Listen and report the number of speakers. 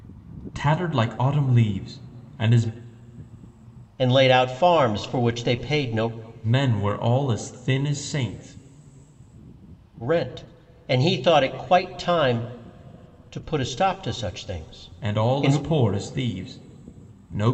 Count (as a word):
two